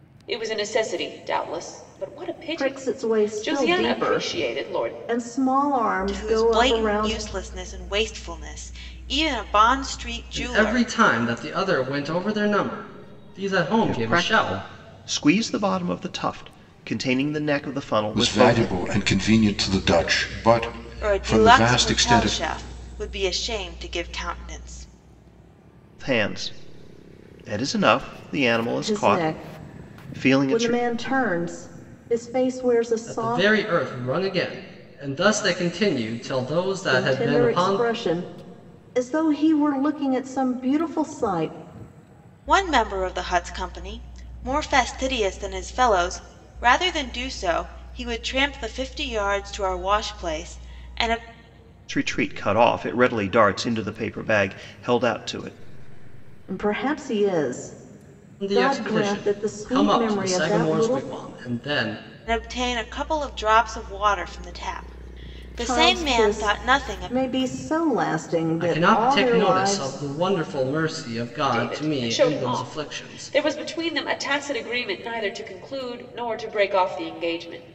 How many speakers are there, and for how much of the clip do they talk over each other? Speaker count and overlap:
6, about 24%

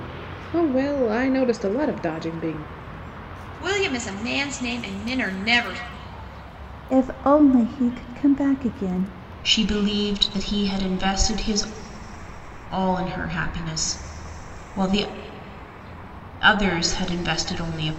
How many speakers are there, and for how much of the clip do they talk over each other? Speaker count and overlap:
4, no overlap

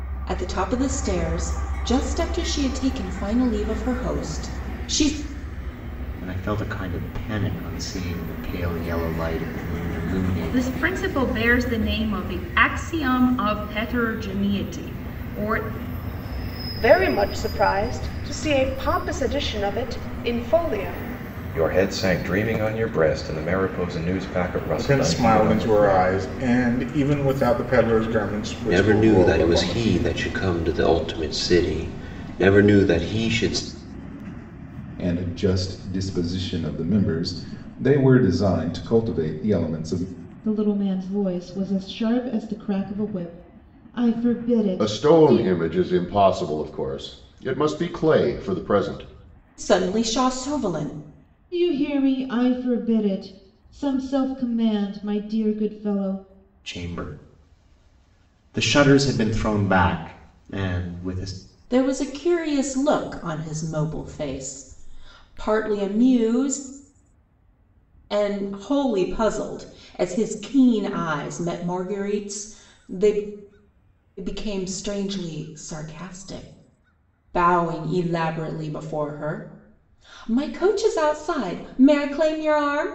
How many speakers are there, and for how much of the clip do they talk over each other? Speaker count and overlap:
10, about 5%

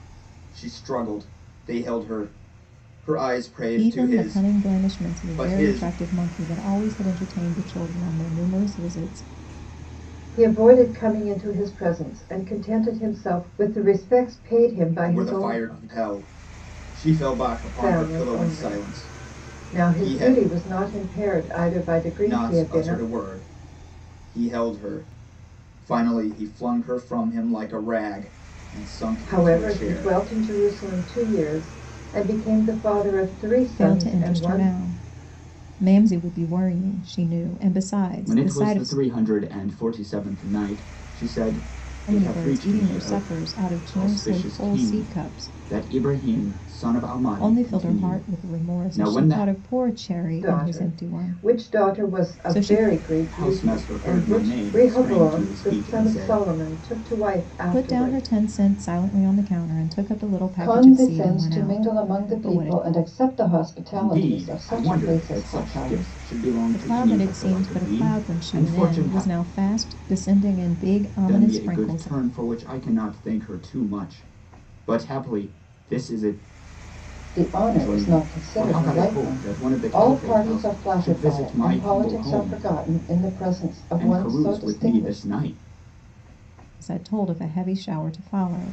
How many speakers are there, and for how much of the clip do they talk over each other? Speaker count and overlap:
3, about 38%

